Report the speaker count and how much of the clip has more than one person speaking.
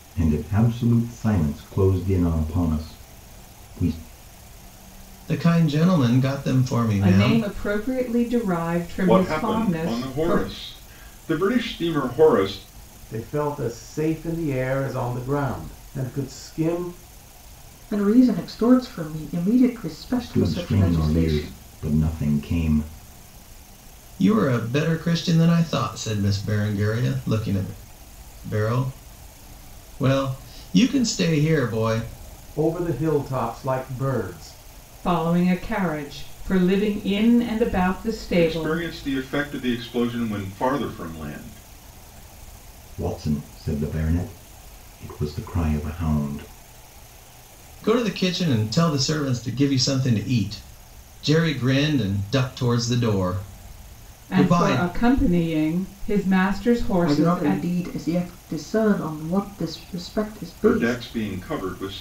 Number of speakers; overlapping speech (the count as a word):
six, about 9%